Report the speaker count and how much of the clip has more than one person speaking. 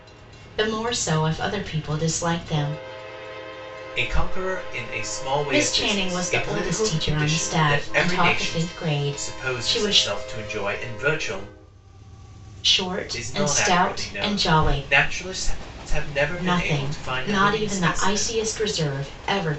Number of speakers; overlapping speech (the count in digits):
2, about 40%